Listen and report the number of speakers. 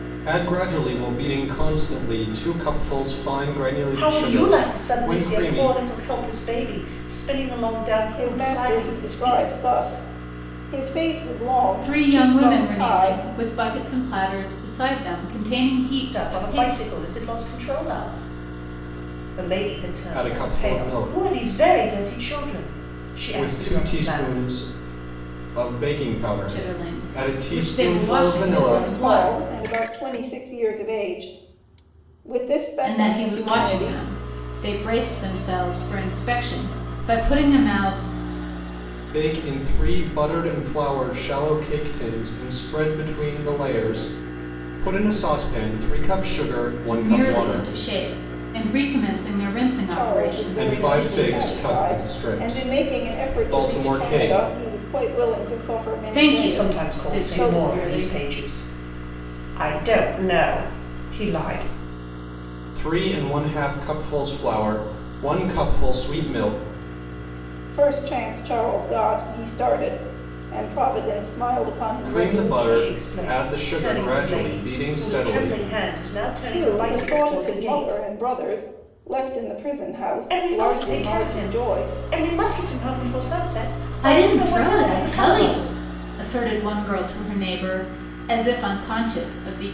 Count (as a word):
four